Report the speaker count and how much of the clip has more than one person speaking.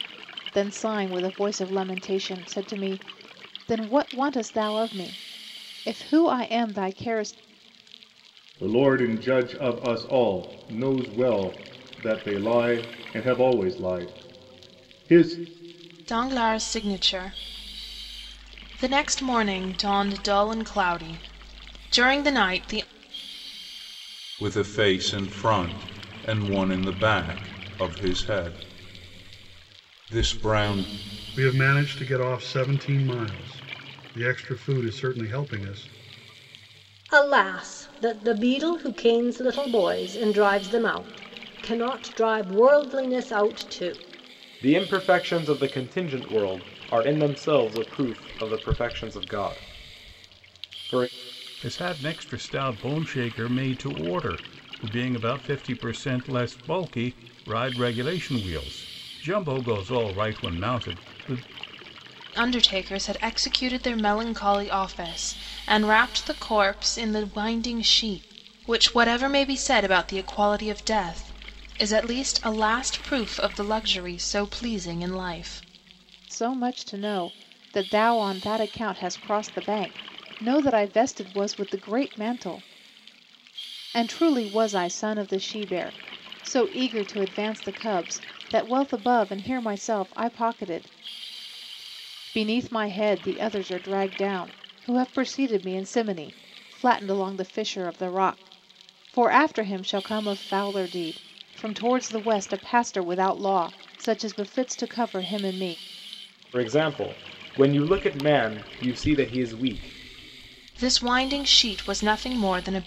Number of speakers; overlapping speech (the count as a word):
eight, no overlap